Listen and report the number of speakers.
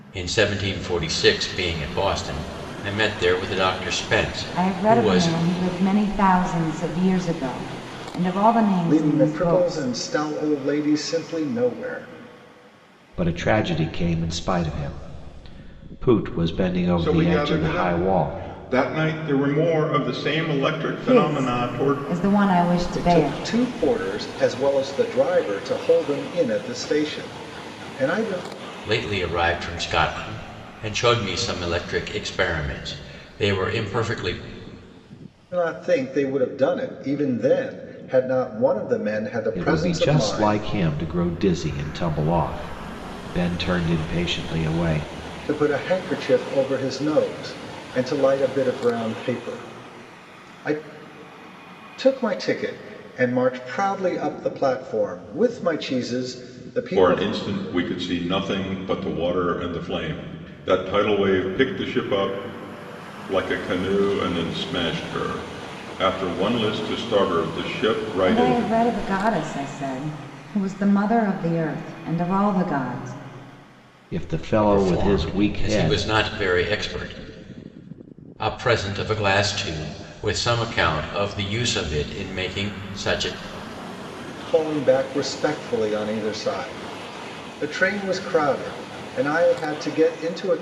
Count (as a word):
five